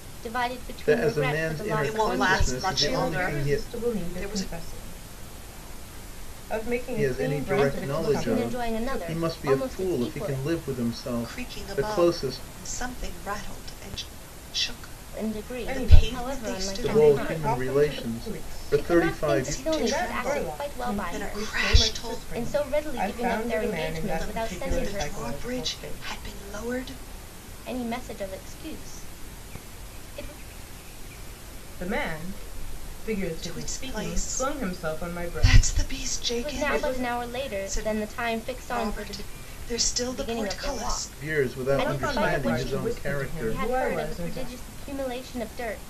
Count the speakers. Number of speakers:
four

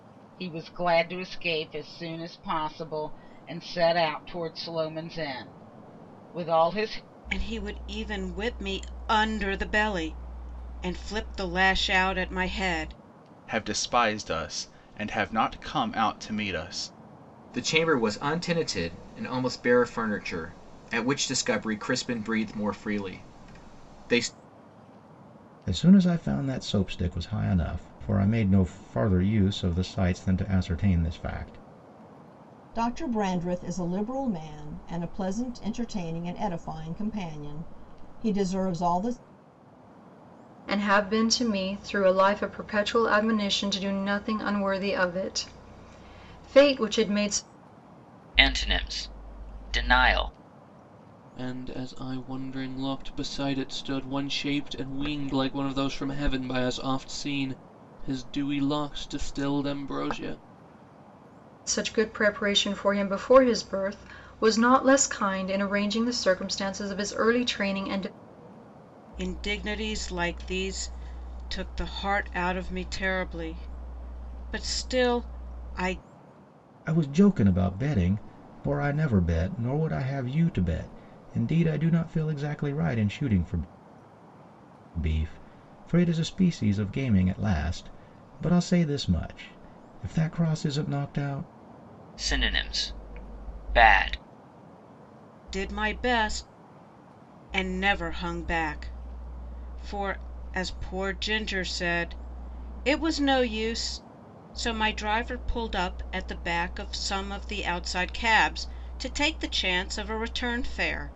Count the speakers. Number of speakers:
nine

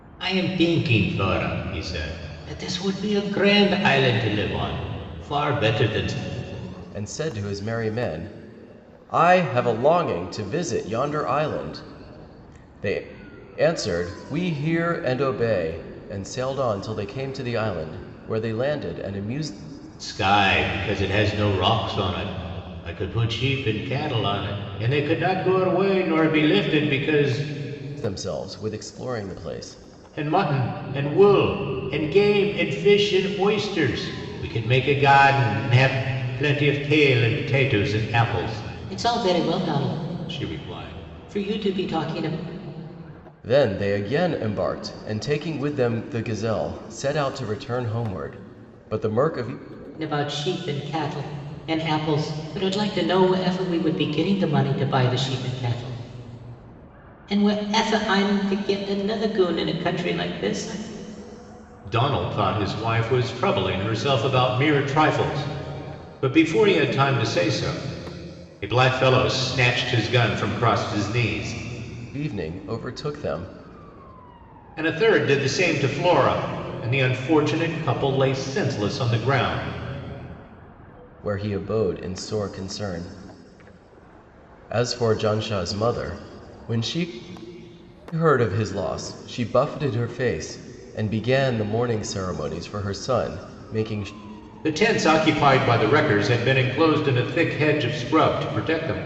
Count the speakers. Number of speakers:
two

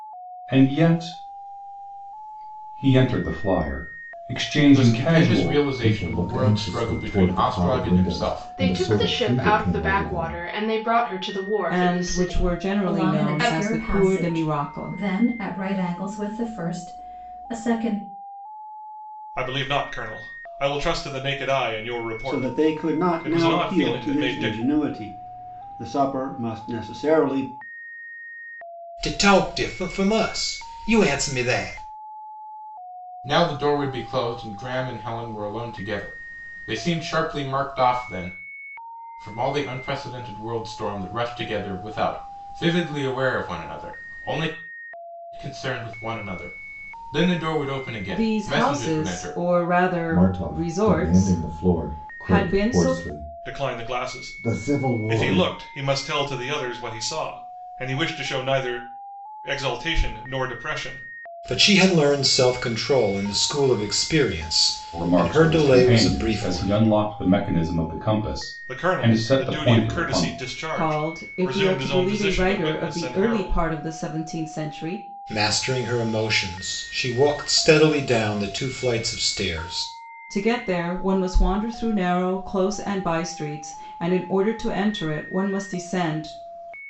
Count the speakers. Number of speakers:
nine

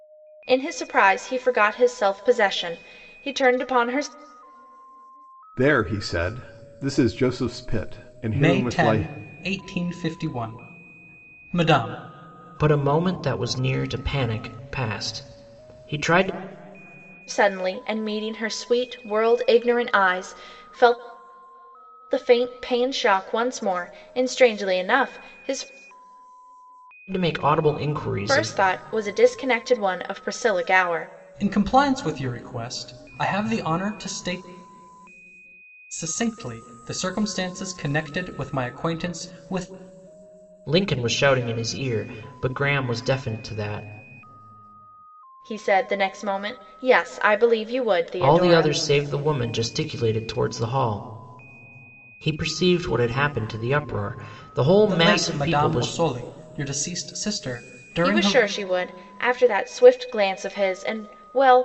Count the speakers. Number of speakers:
four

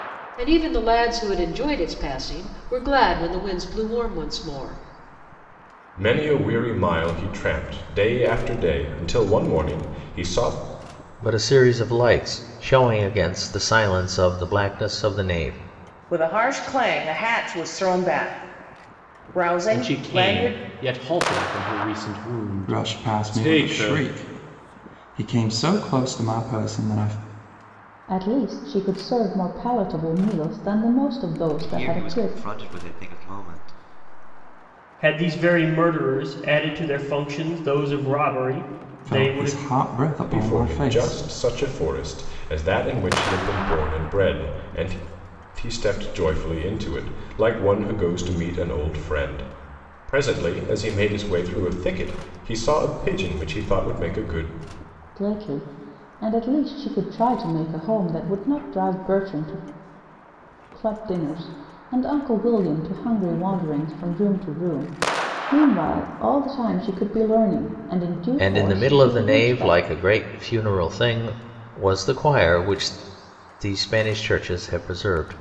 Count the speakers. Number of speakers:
nine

